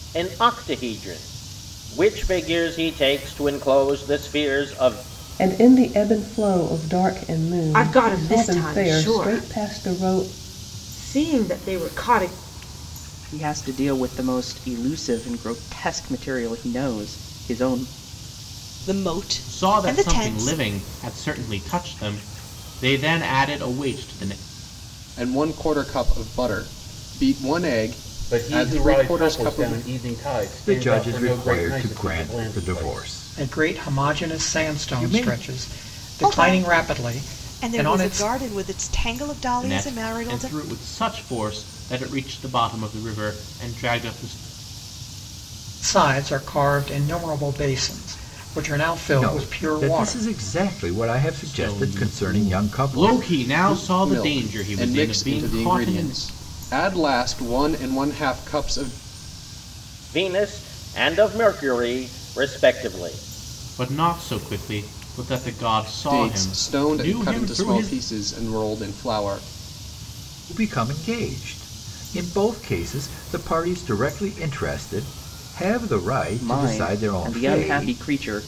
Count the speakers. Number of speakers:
10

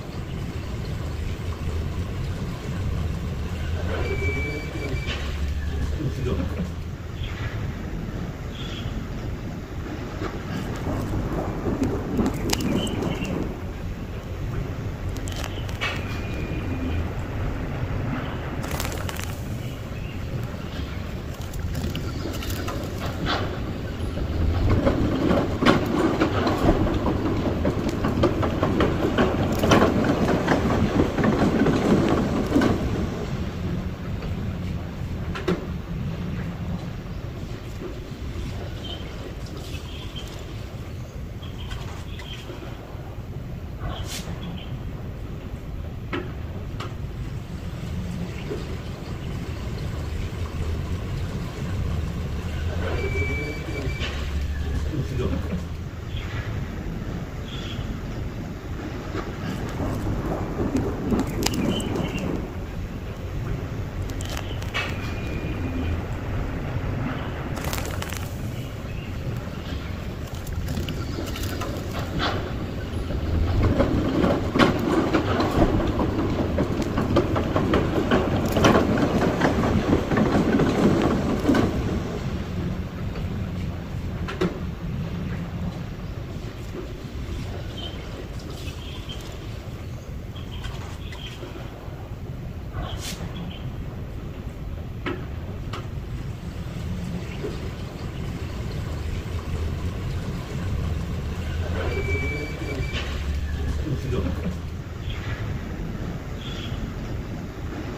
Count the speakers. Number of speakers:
0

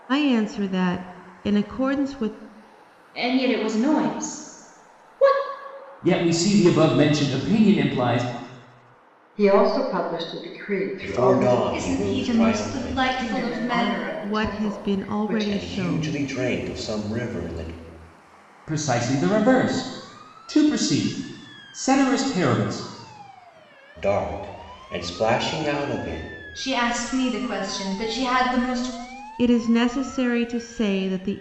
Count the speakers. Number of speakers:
6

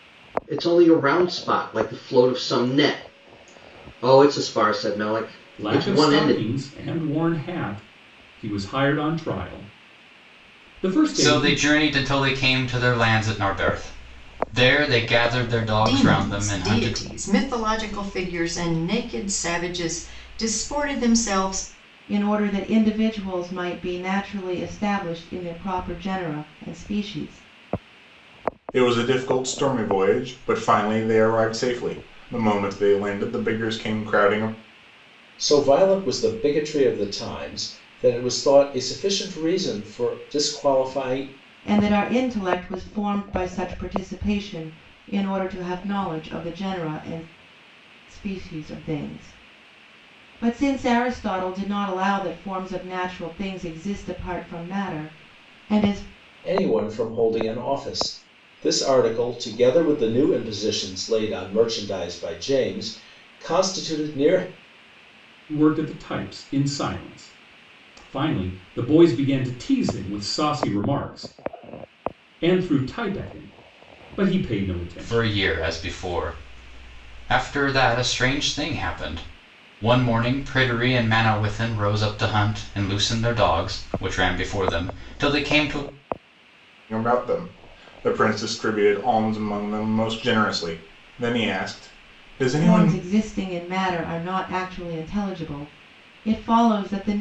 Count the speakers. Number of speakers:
7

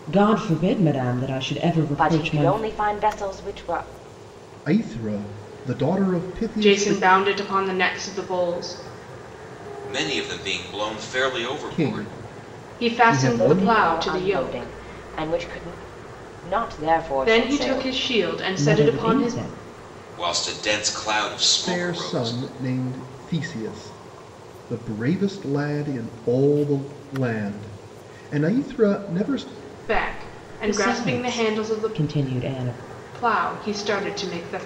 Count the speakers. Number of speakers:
5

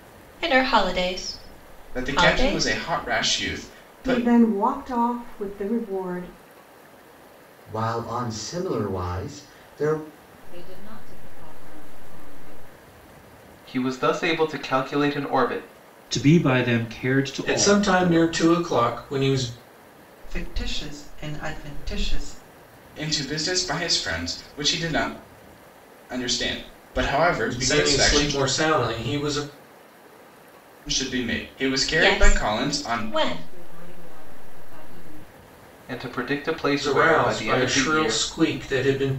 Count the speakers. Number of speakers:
9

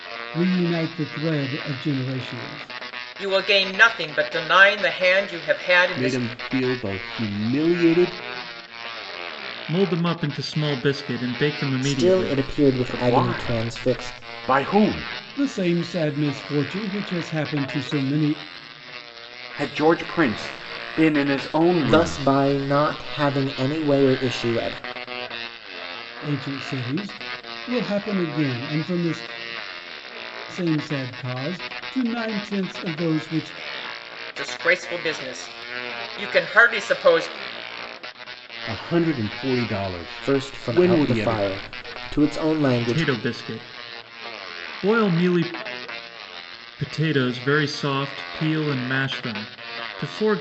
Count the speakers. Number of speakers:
6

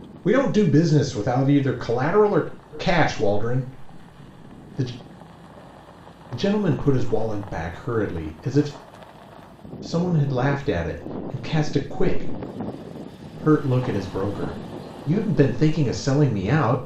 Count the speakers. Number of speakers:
1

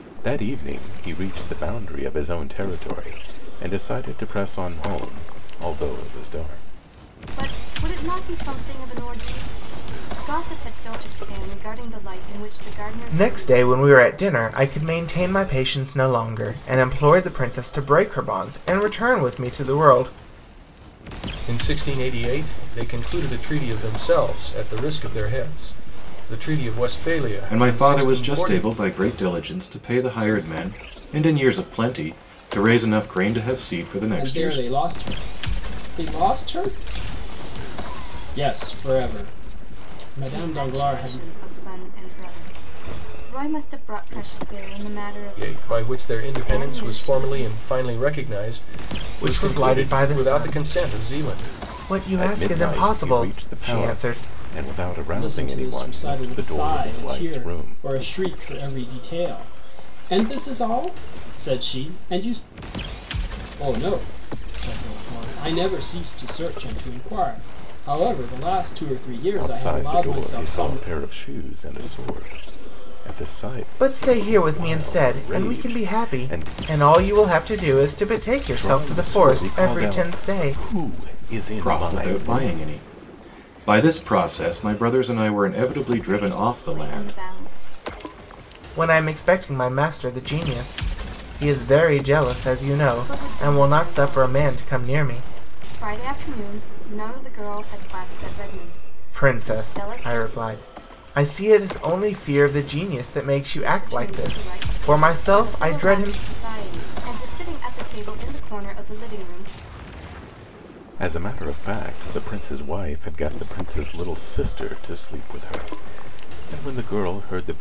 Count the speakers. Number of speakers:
6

